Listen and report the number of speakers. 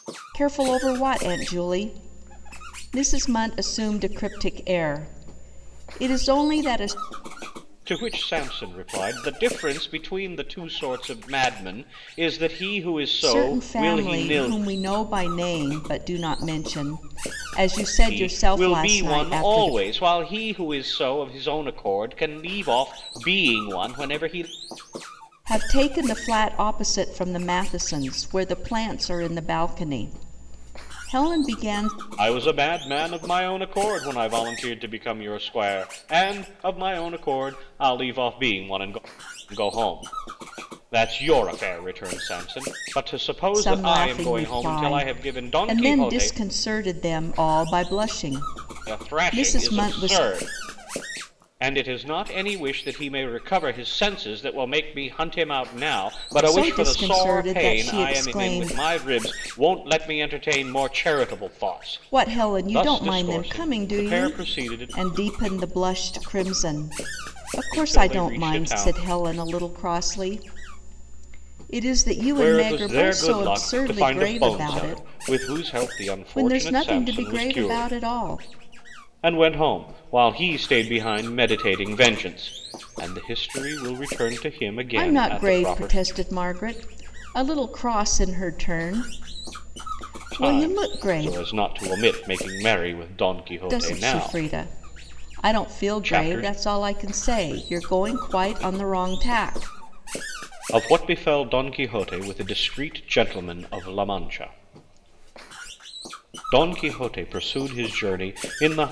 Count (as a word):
two